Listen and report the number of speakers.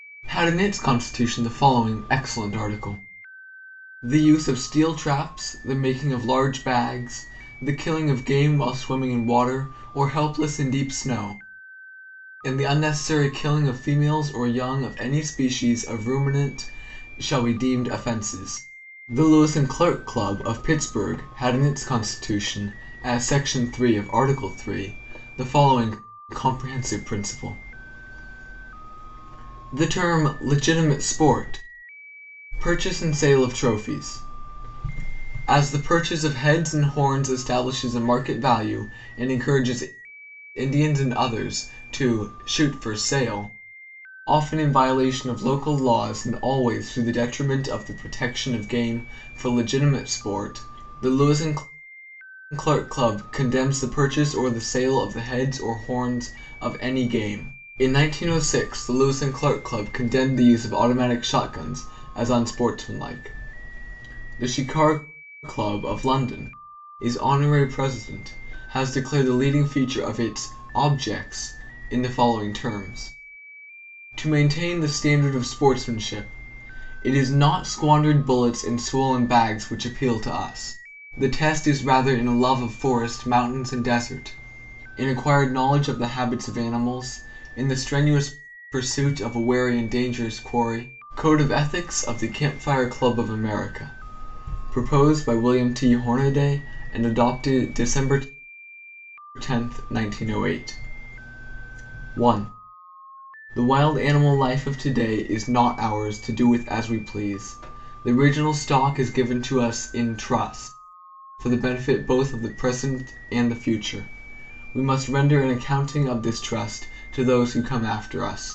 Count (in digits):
1